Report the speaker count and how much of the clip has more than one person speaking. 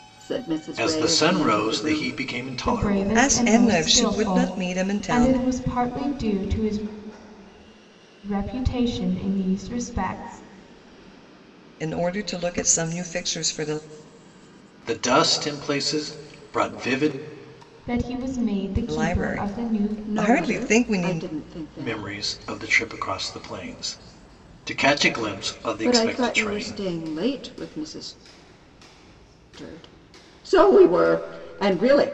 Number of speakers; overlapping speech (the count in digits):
4, about 23%